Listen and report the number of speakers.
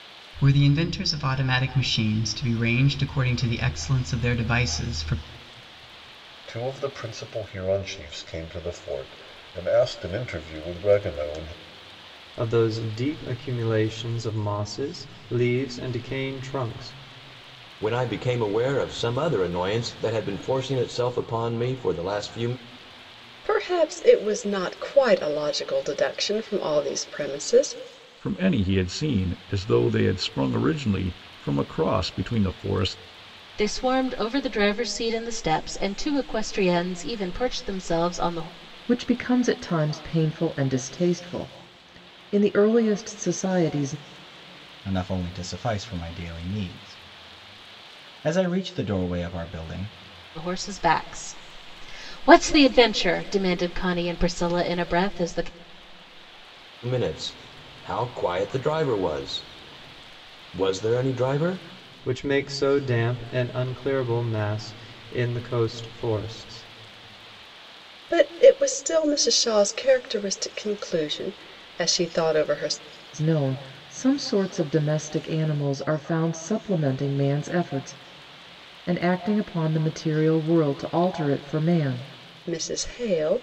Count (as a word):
nine